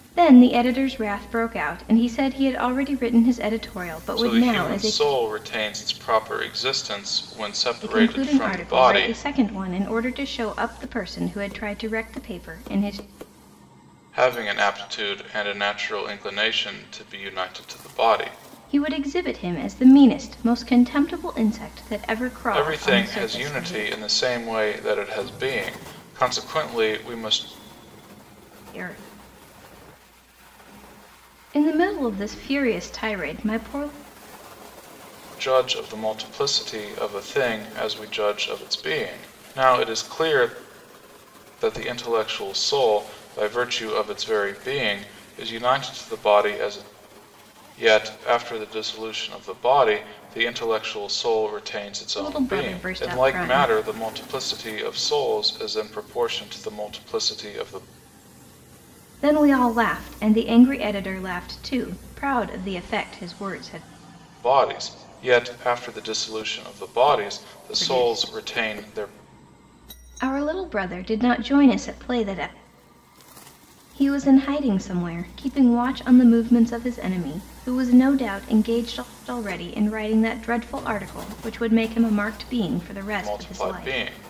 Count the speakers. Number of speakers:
two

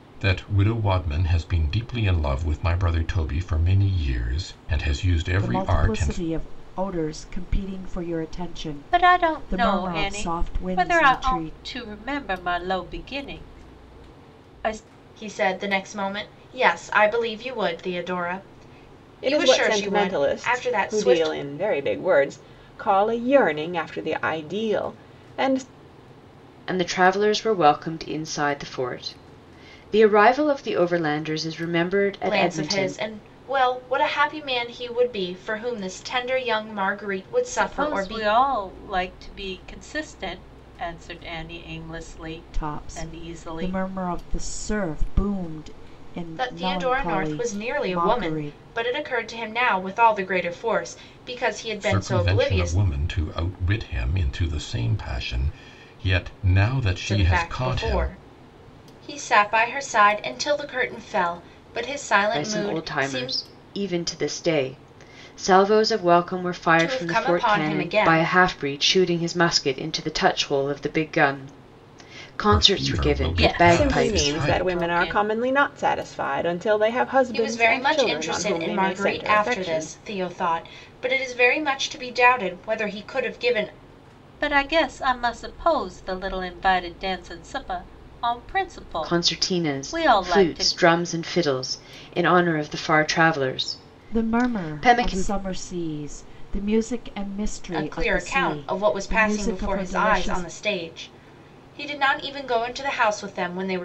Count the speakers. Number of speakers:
six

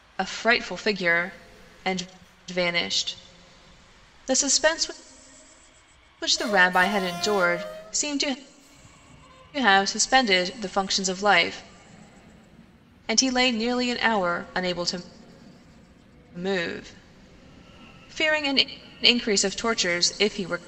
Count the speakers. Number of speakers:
one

